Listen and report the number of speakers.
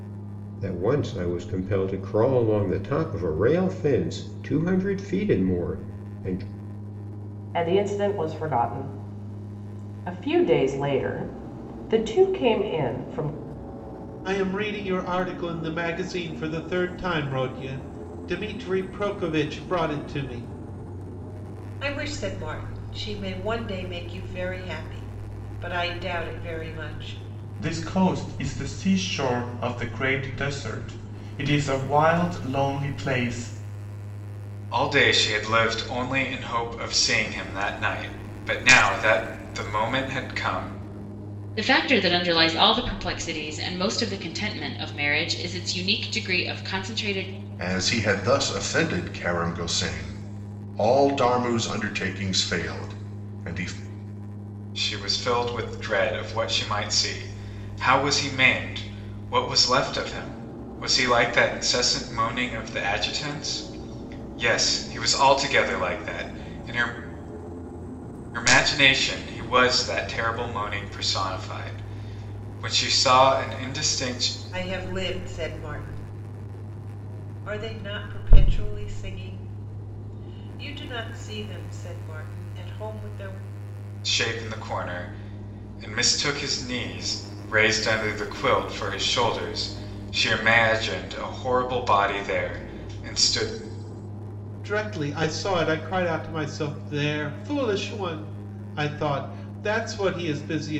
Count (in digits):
8